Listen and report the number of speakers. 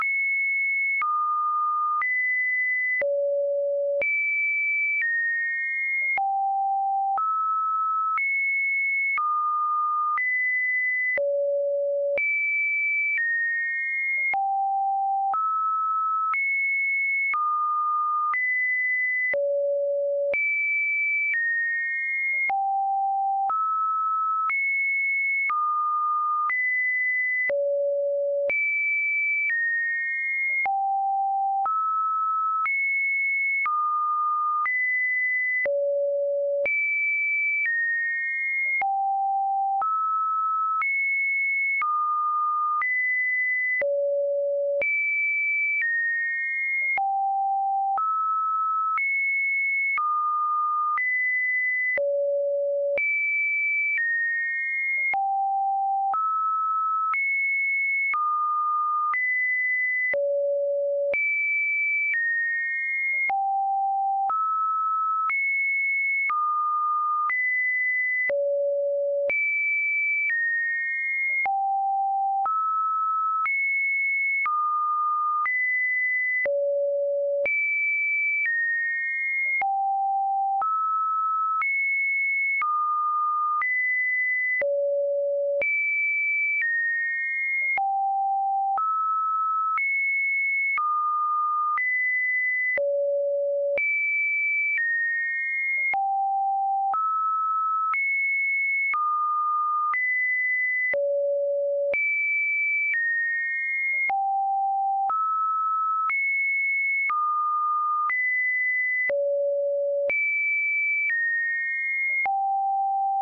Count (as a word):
zero